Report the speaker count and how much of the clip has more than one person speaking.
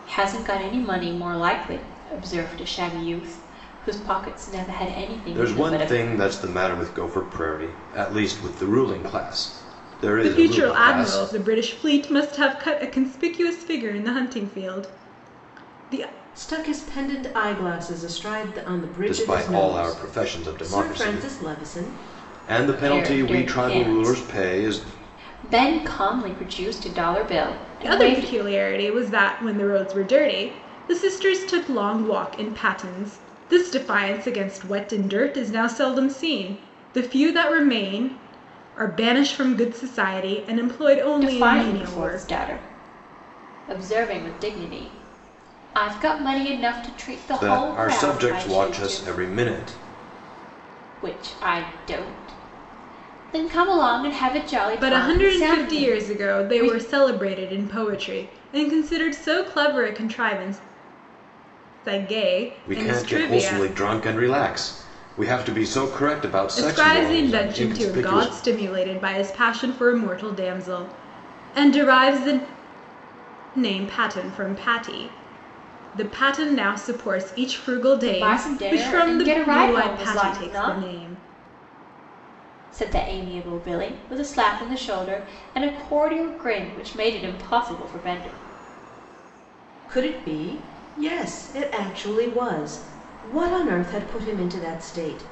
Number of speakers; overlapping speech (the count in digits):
4, about 19%